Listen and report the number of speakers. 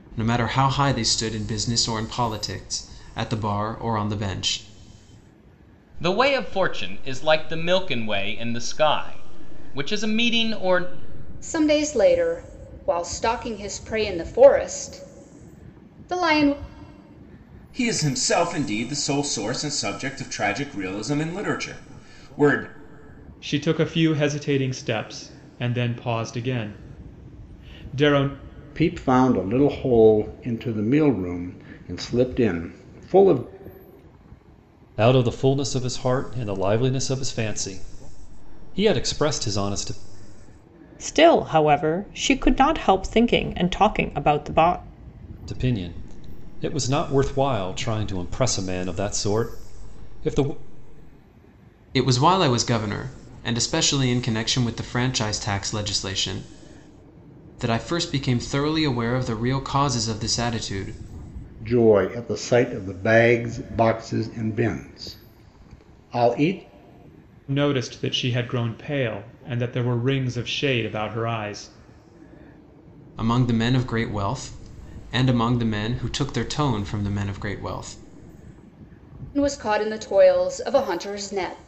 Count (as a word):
eight